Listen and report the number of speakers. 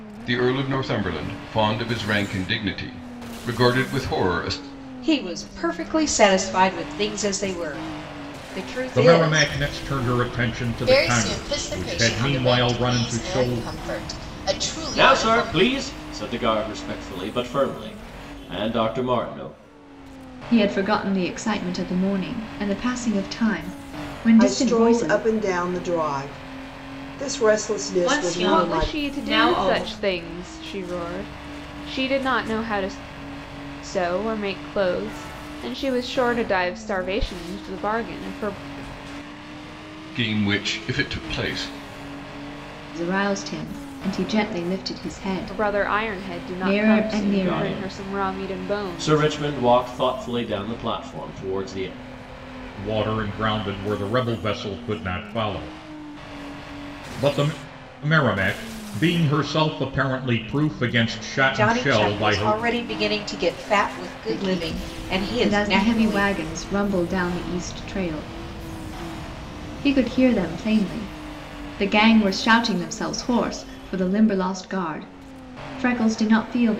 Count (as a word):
nine